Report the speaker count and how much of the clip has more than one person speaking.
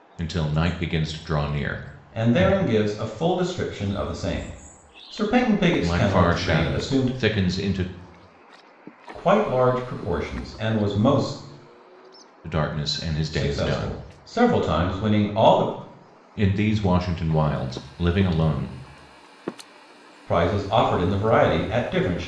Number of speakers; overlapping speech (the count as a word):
two, about 11%